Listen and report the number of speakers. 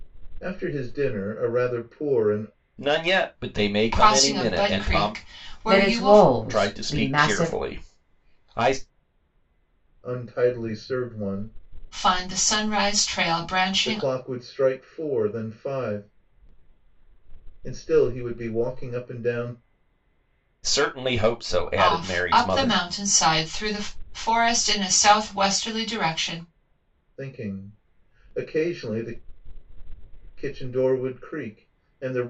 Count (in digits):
4